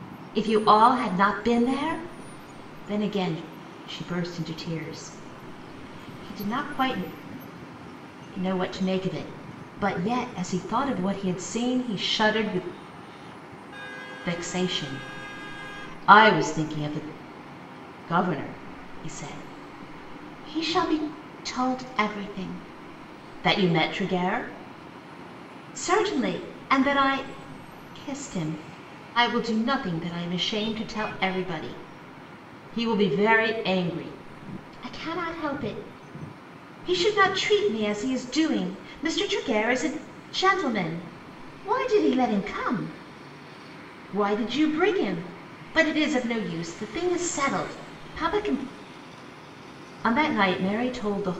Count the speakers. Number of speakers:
1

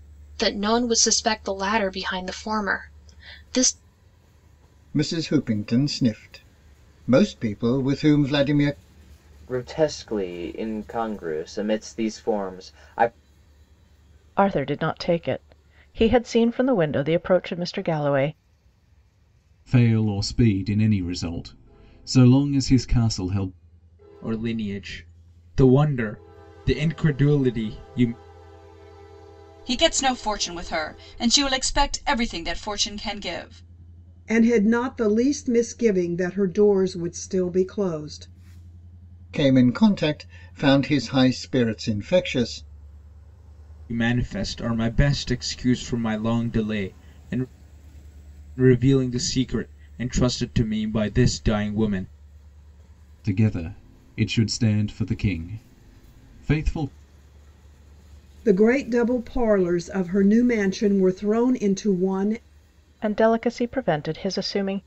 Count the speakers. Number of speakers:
8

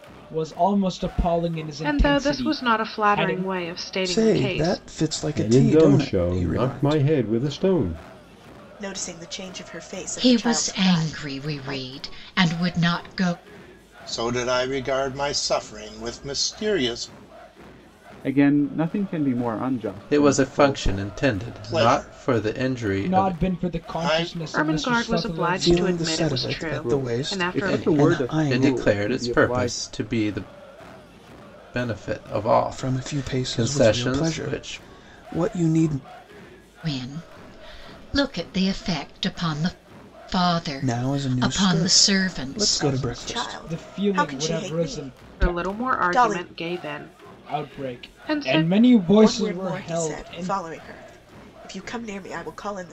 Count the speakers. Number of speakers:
9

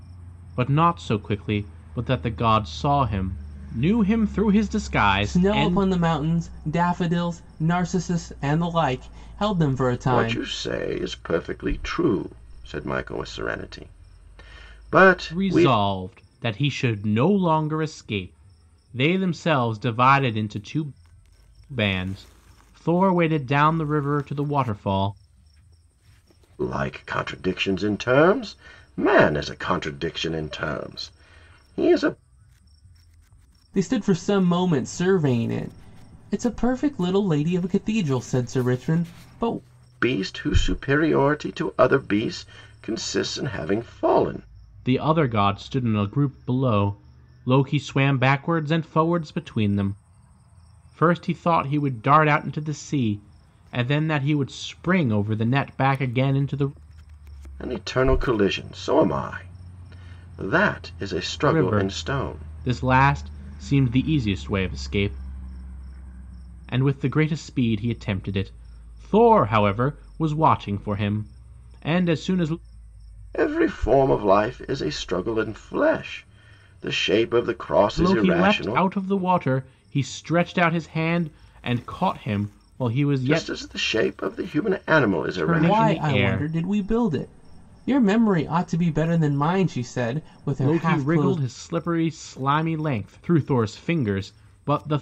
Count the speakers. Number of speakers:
3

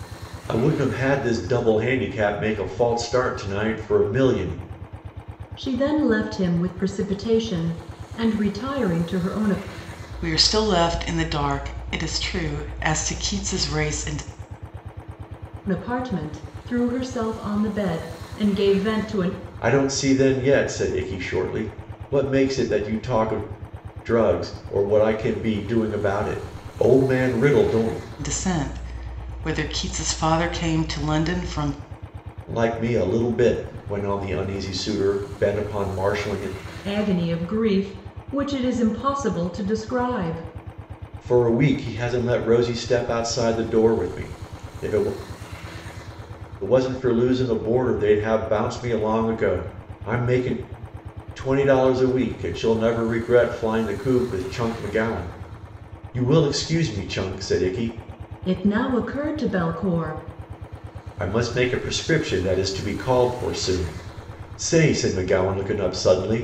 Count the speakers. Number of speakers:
3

